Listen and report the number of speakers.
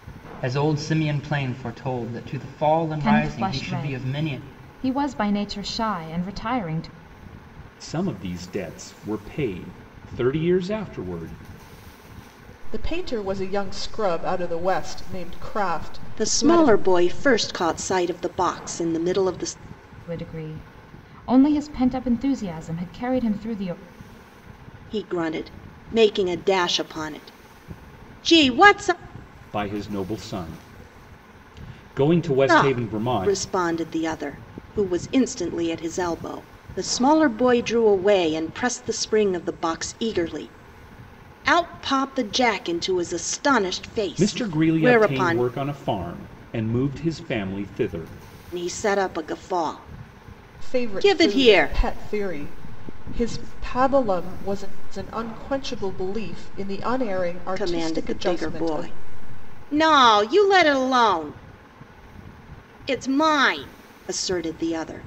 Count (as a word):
five